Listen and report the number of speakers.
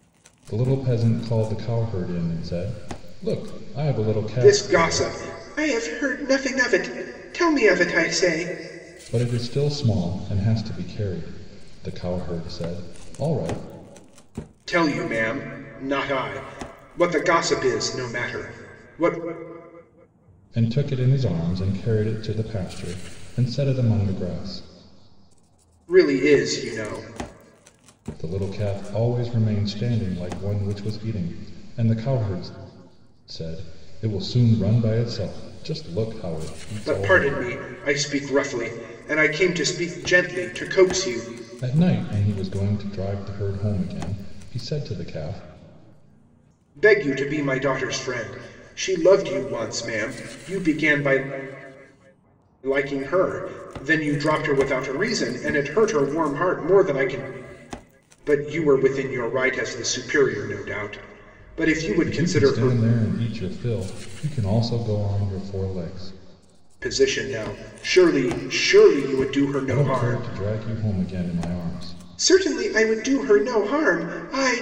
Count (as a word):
two